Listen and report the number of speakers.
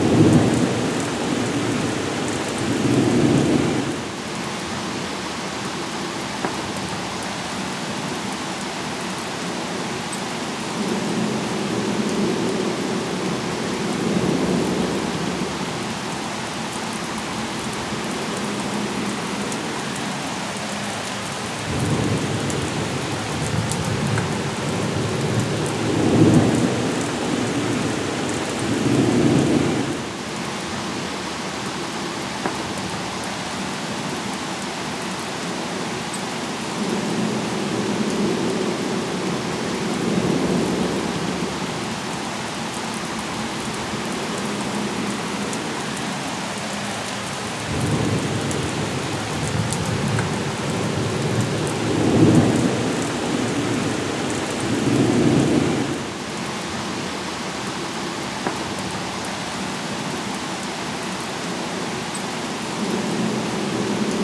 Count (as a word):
zero